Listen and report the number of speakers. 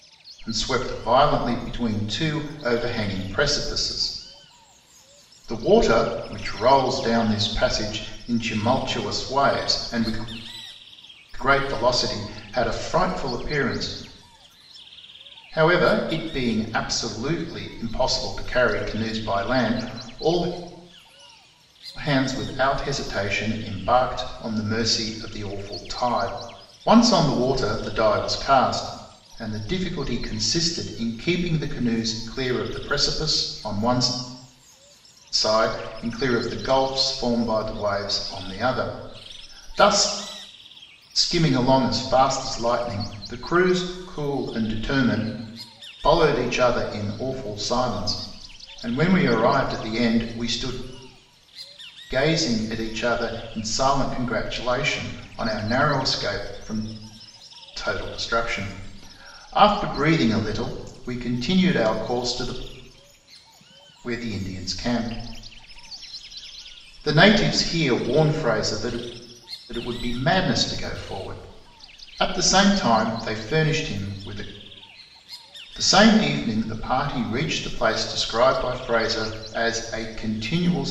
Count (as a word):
one